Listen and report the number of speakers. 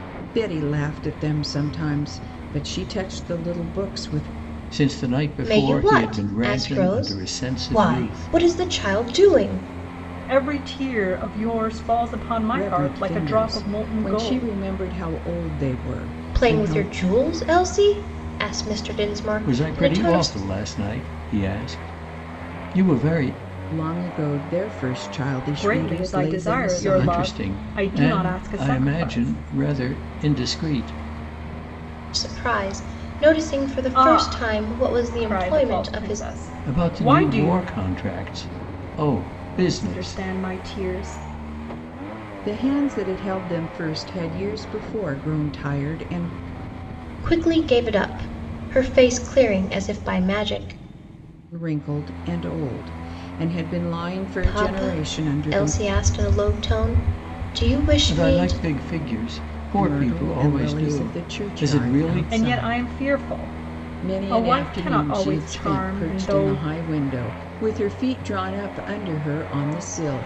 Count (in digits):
4